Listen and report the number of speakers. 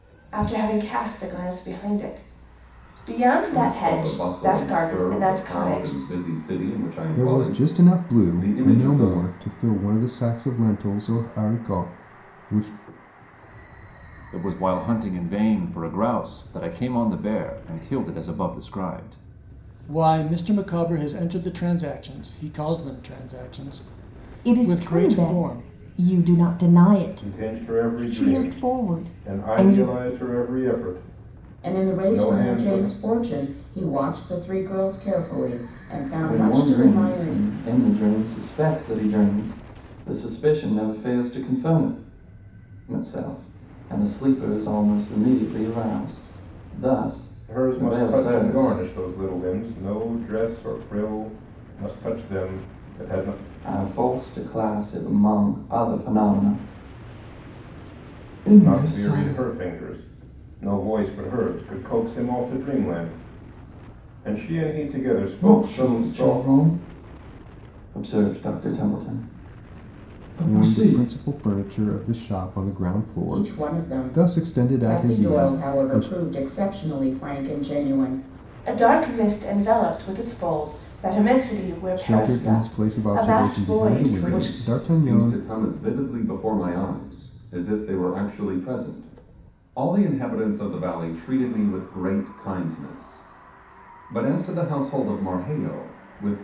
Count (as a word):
nine